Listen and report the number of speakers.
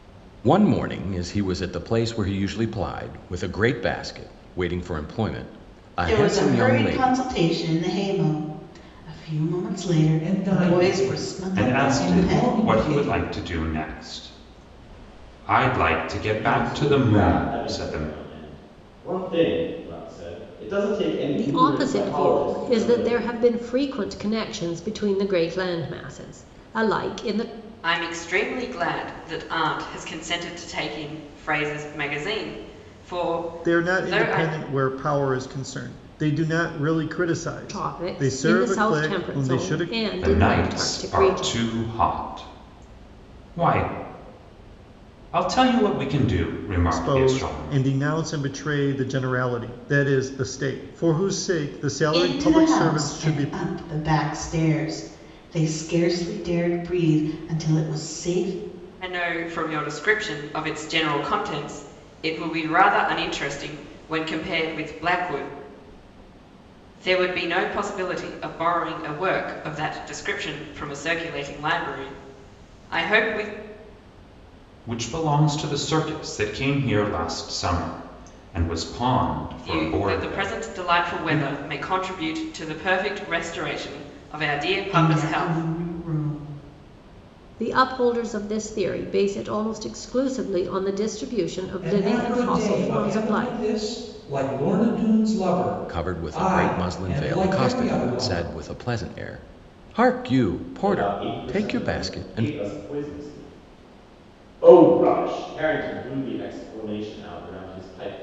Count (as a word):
eight